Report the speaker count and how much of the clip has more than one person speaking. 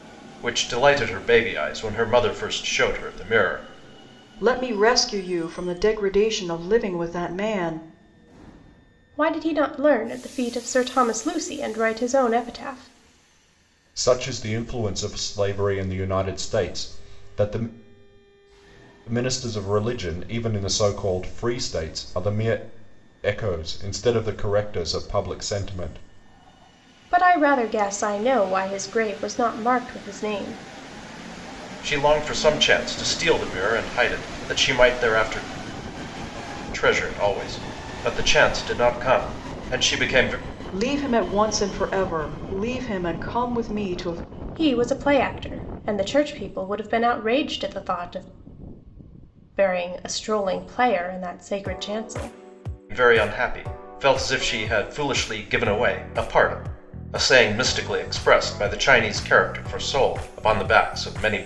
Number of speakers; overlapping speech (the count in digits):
4, no overlap